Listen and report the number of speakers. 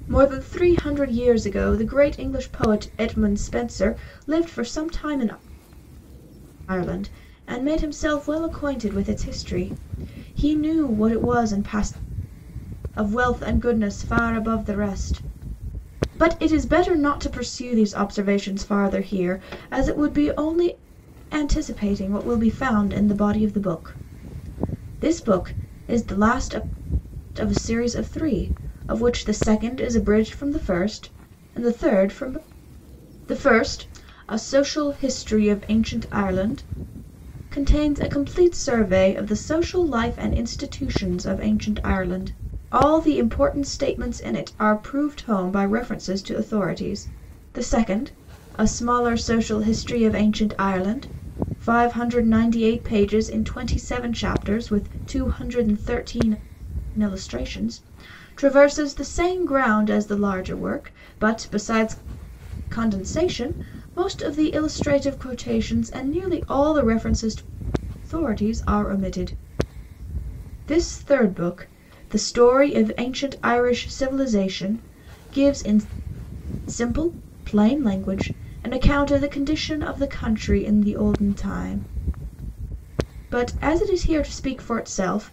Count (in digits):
1